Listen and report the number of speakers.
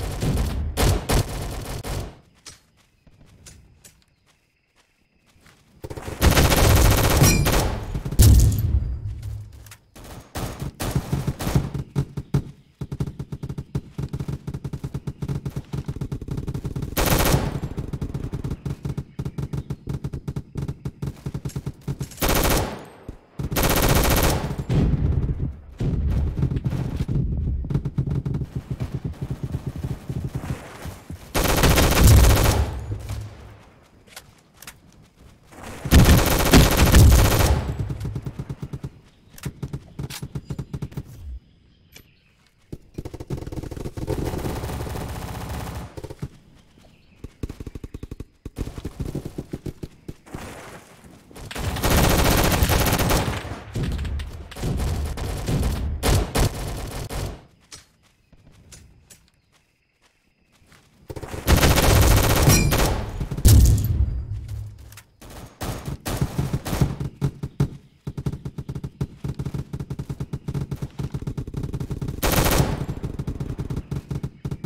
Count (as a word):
zero